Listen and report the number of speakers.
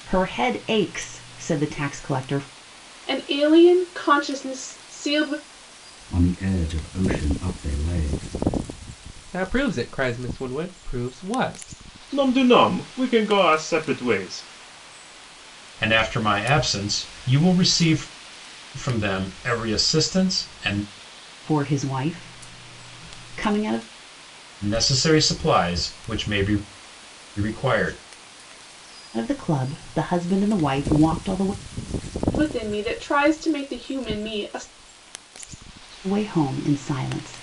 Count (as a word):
six